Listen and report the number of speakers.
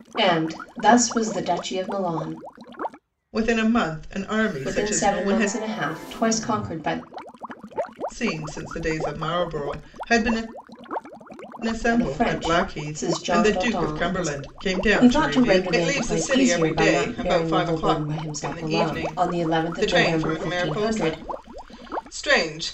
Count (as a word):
two